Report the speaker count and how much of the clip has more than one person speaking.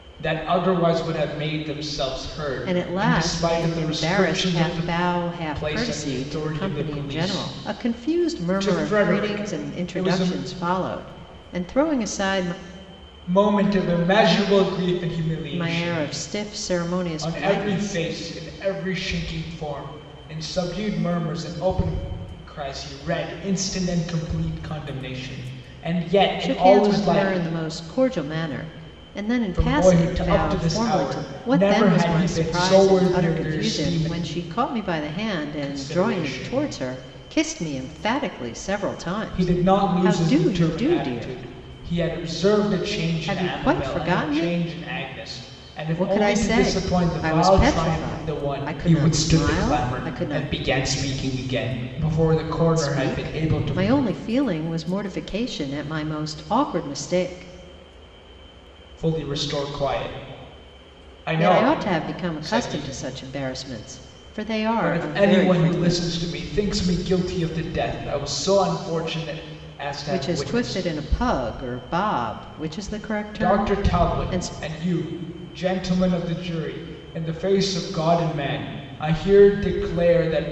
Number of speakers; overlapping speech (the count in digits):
2, about 36%